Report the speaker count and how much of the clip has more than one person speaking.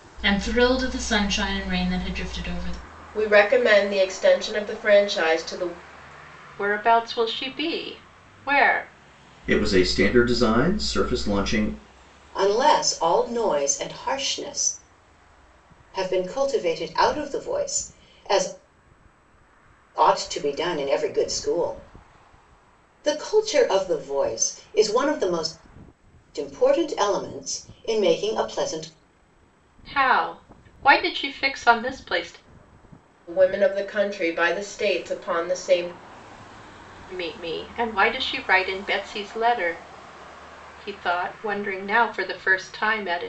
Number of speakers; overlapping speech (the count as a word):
five, no overlap